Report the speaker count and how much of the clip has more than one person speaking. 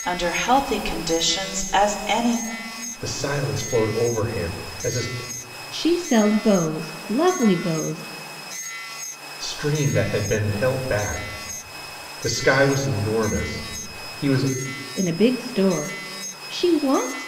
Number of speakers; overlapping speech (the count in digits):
3, no overlap